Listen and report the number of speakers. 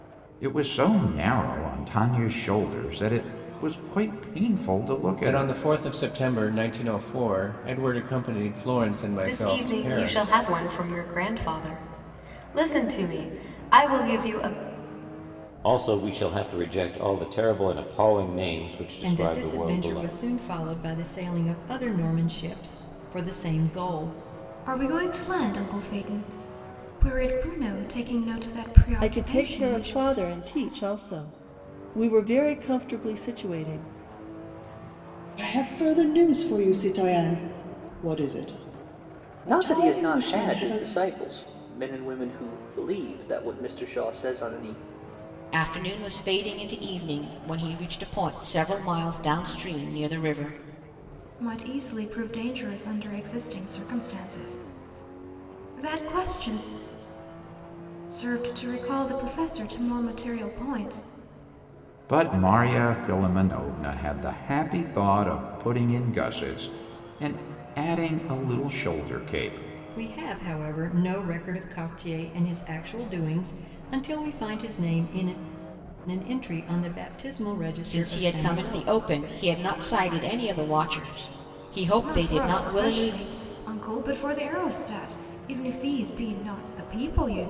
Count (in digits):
10